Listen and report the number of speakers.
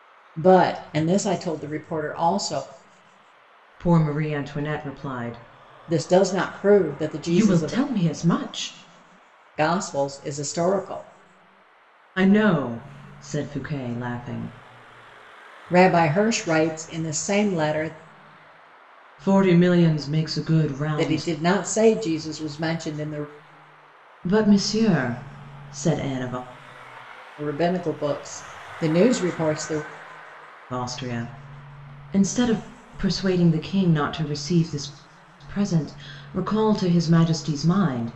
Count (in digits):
2